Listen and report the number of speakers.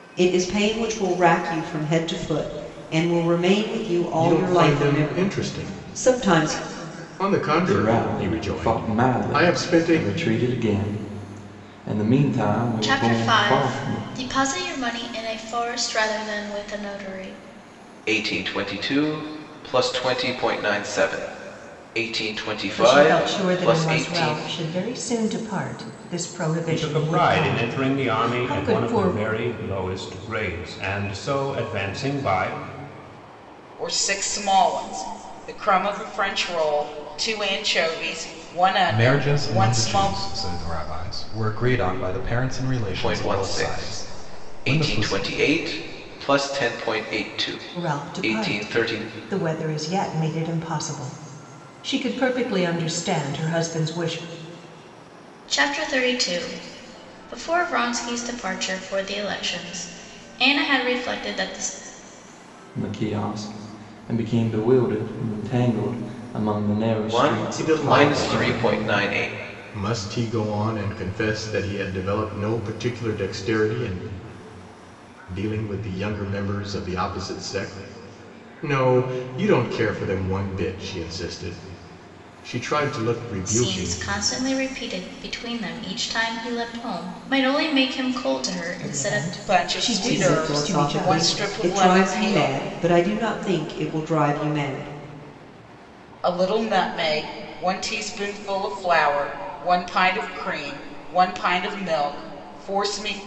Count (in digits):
9